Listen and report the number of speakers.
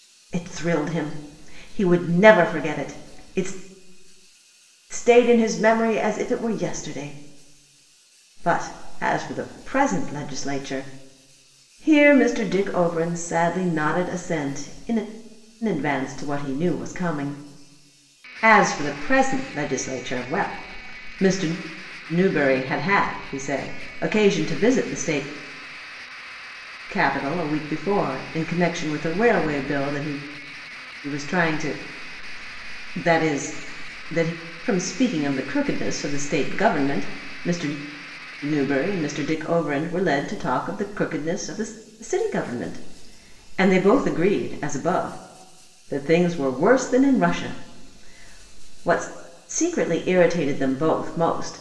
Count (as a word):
one